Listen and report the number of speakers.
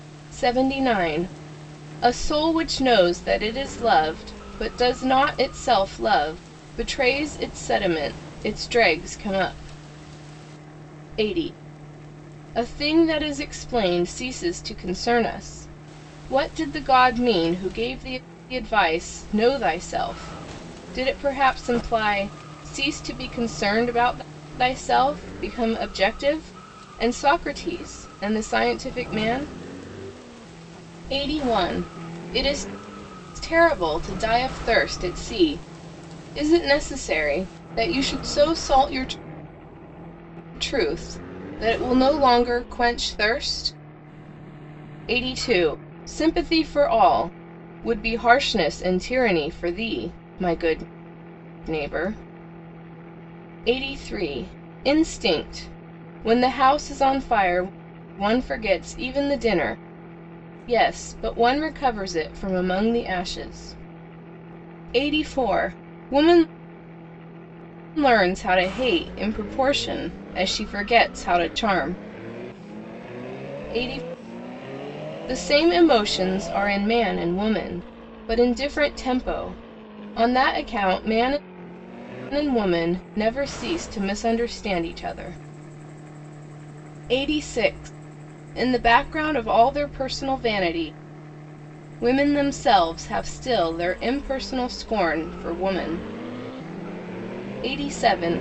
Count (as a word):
one